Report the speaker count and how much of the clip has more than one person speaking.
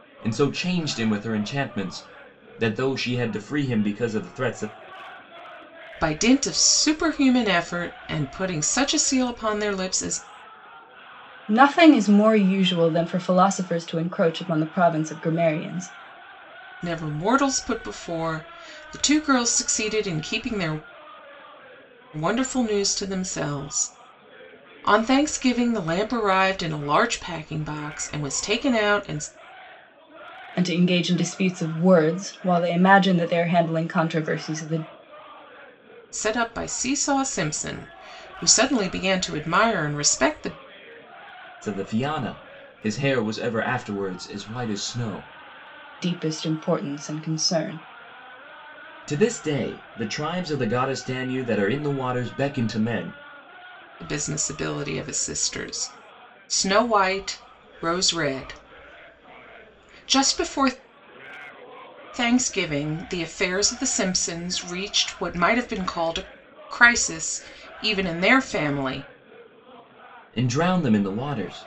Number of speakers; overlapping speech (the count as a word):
three, no overlap